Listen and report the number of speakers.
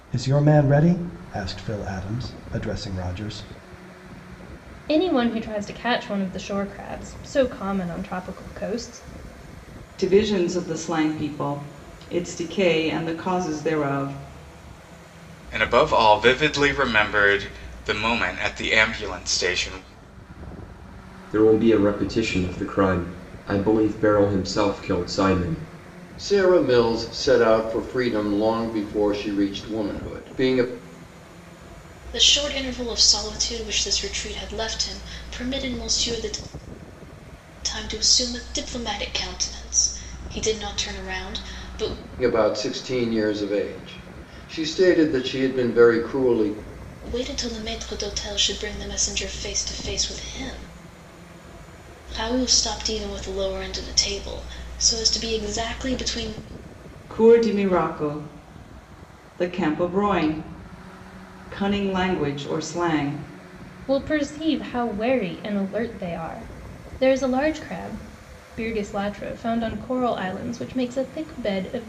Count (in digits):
7